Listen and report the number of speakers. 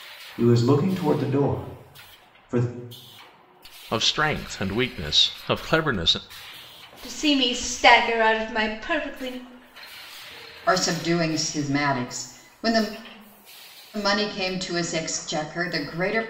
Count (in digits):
4